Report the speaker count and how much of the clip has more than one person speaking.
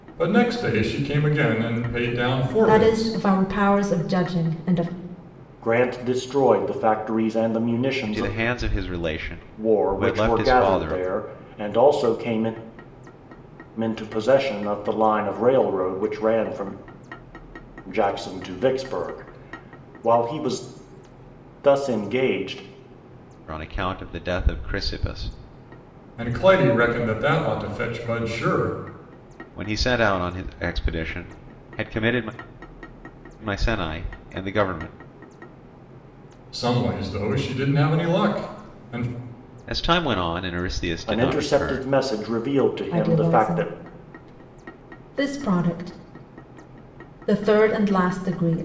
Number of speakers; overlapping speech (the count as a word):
four, about 9%